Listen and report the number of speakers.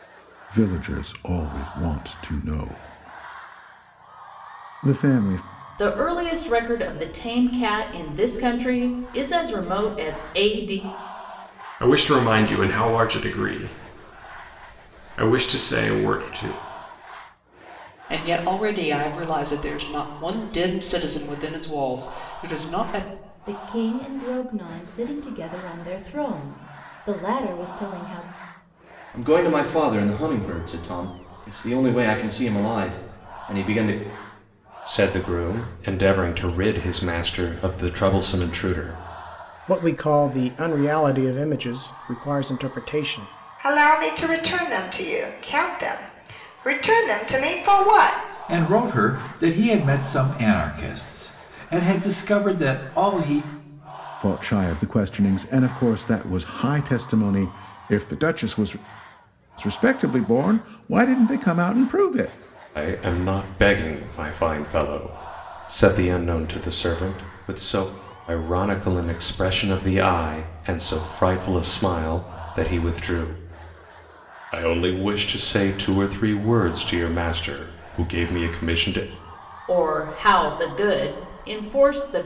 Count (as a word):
ten